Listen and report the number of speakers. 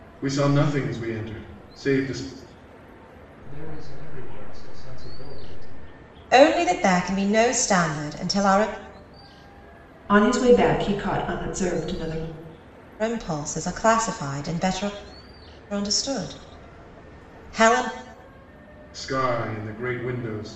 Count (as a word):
four